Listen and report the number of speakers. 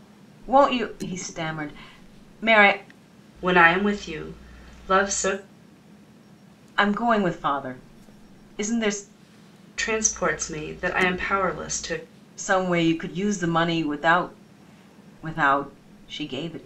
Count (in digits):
2